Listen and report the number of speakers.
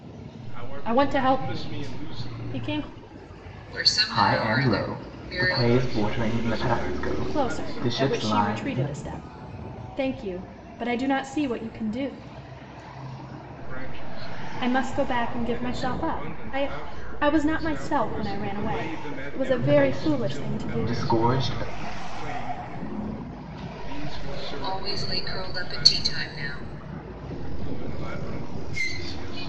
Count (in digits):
4